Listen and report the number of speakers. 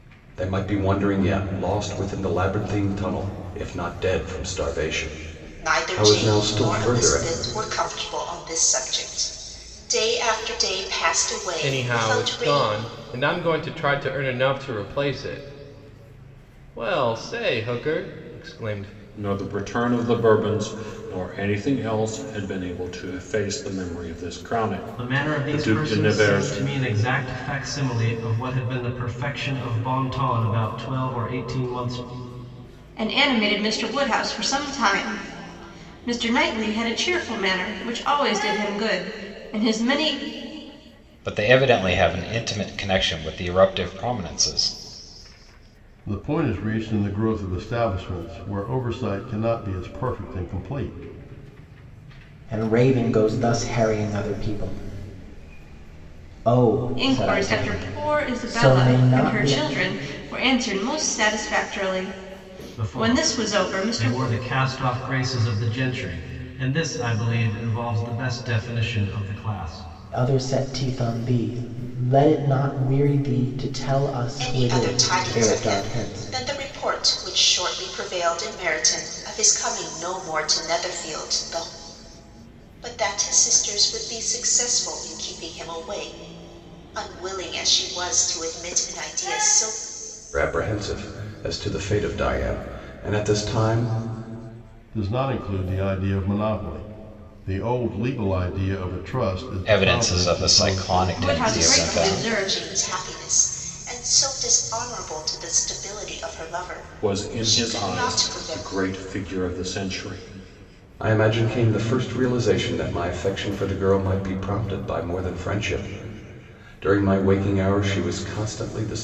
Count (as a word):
nine